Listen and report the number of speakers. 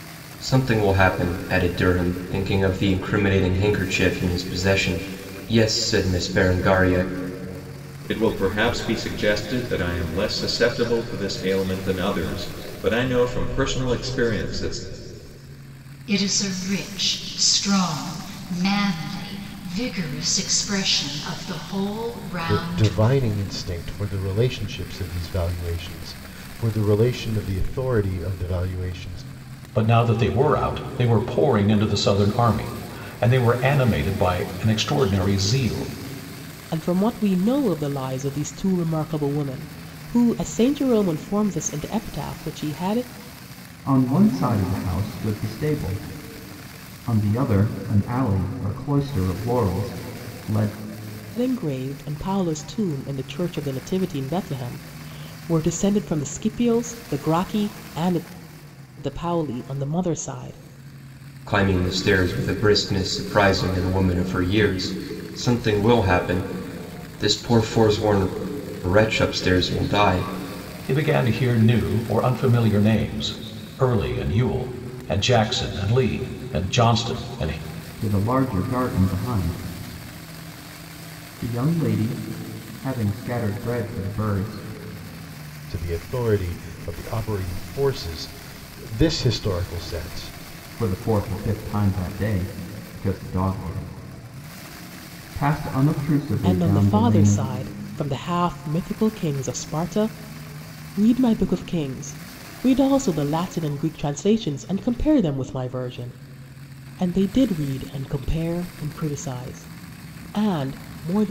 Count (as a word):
seven